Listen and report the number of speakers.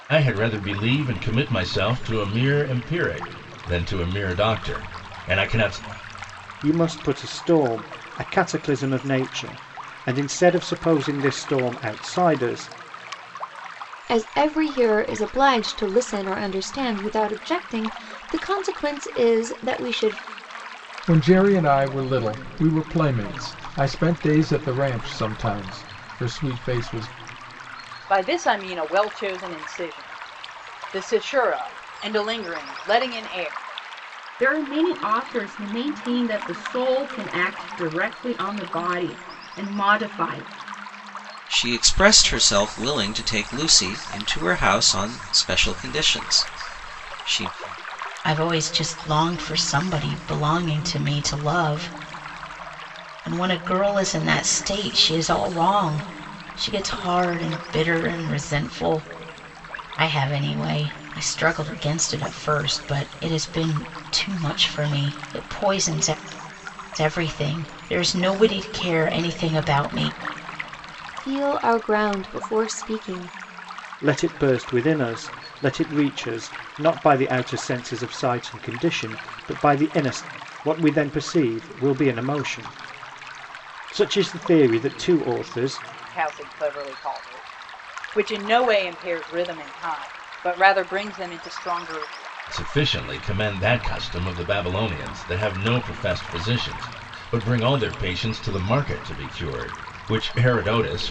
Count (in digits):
8